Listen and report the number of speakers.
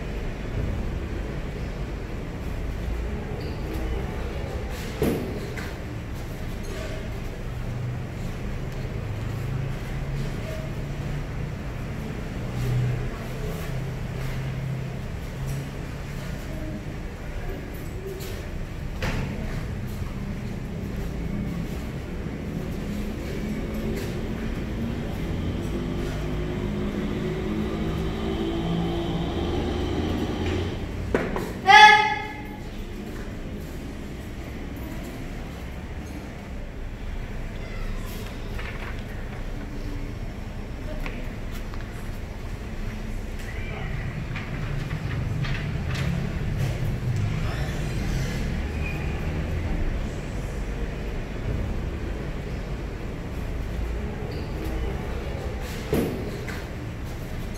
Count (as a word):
zero